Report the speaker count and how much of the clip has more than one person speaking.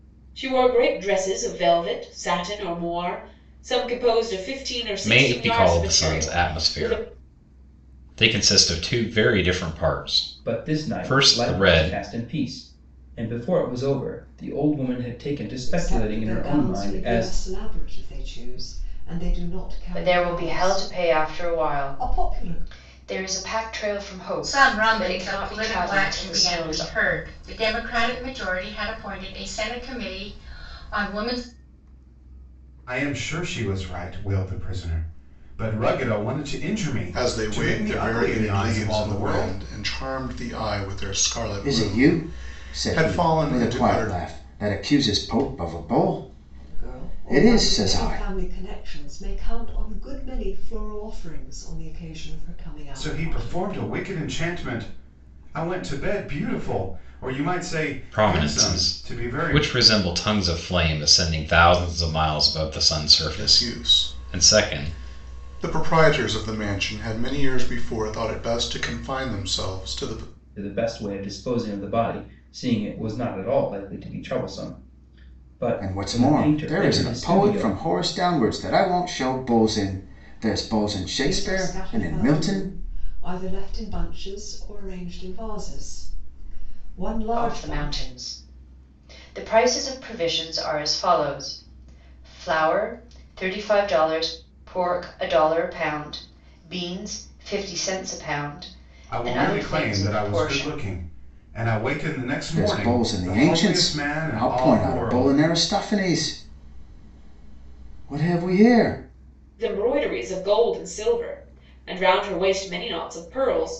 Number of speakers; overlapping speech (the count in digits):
9, about 26%